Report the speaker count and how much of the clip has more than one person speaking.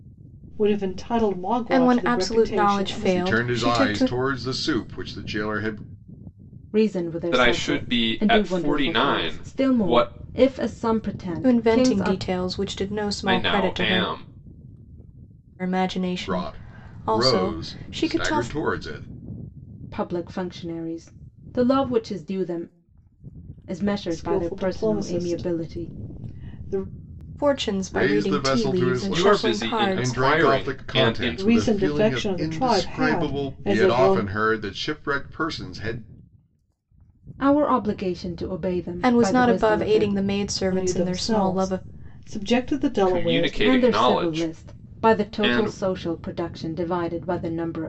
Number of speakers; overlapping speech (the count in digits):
5, about 47%